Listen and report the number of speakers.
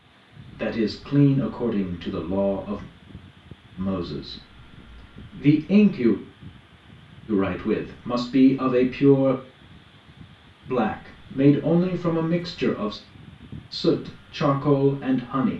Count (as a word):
one